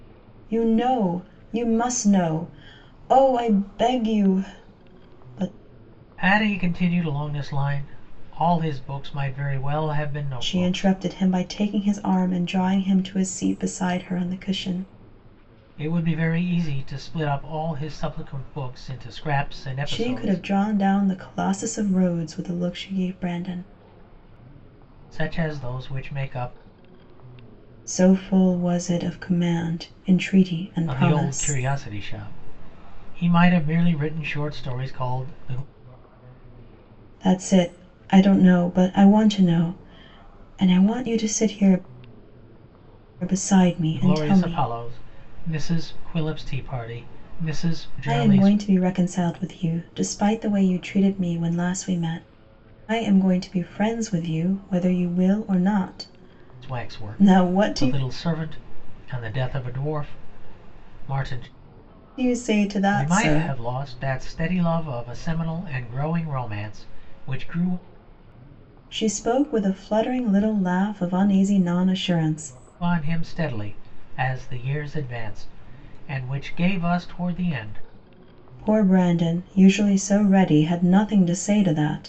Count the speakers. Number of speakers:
2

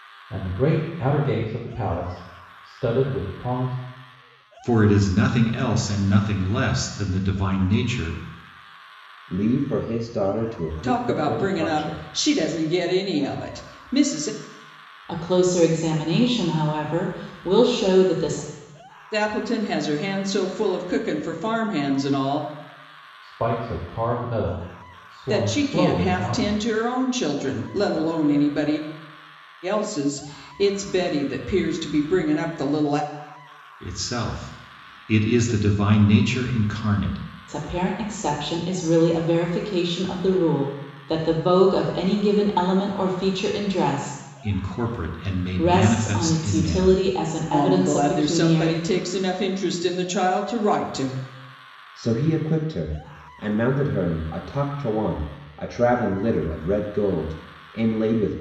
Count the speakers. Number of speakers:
5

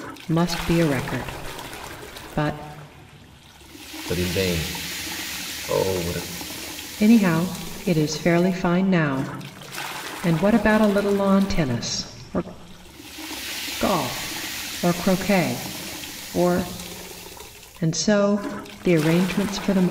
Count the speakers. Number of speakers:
2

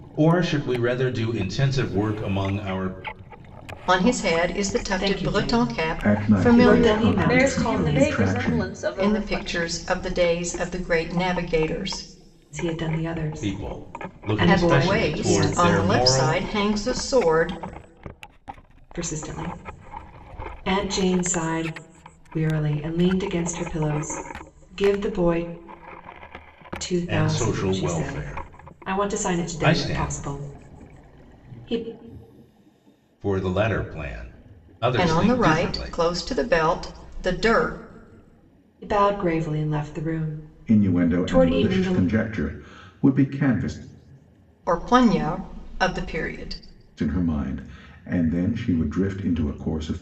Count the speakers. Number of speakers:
5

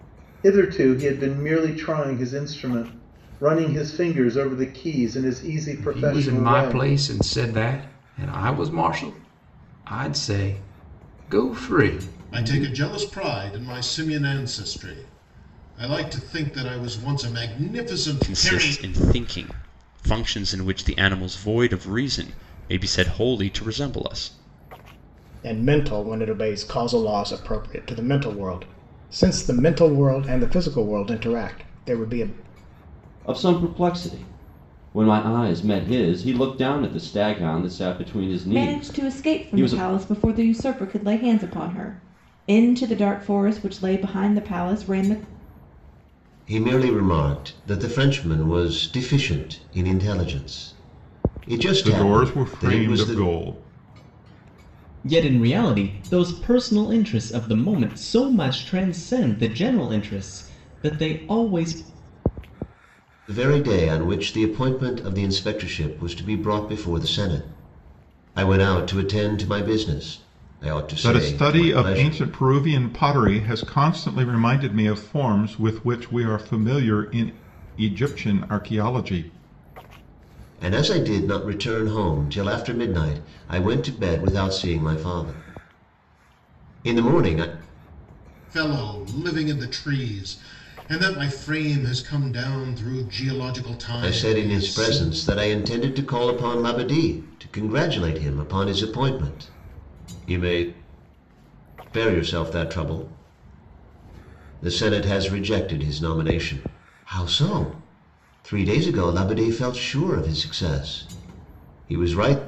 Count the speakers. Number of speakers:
10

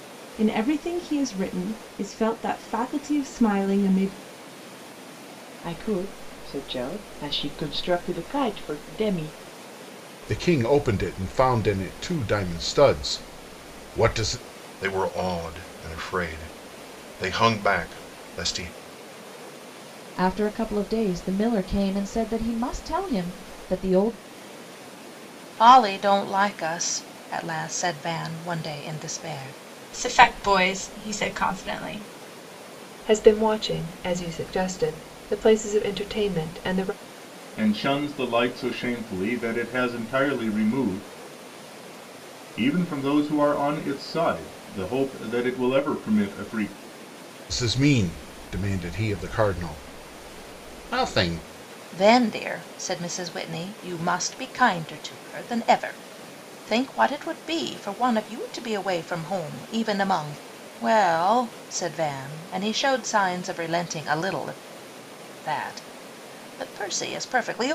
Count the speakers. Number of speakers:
9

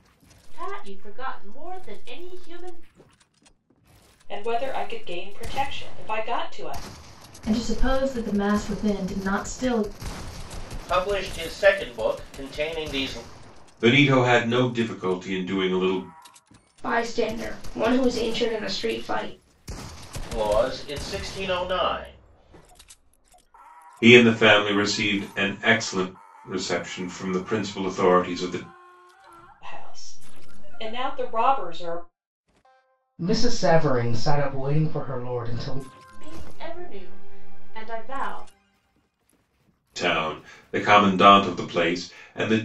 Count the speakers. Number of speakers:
6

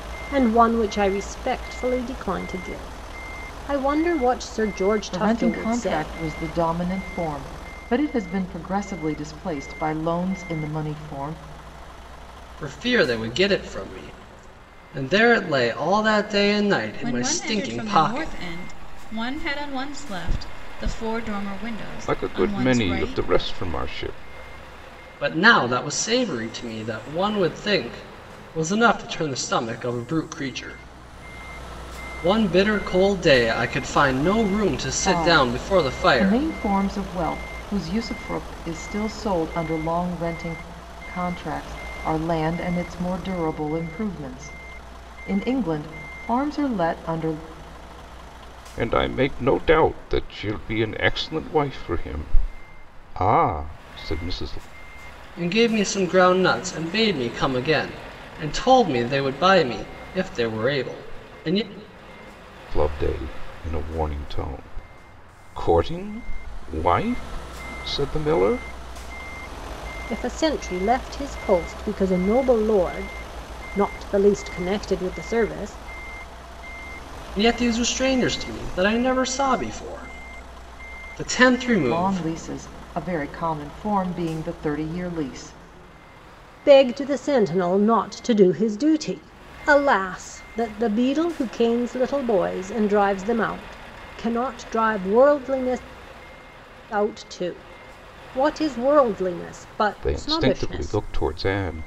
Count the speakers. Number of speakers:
5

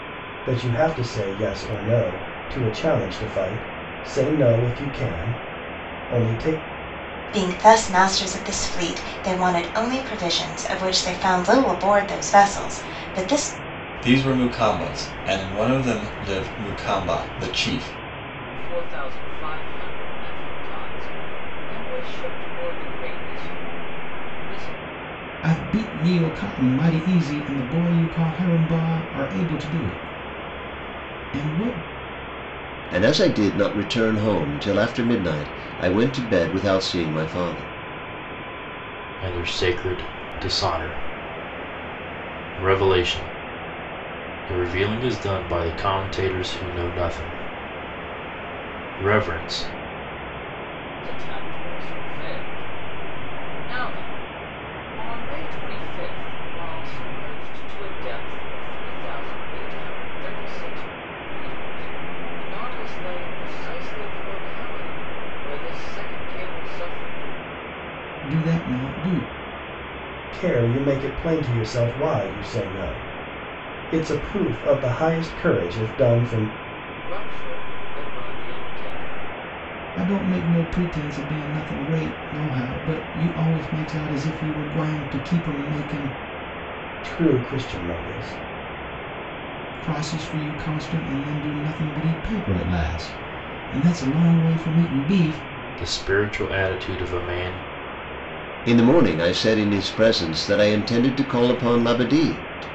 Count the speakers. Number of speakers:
7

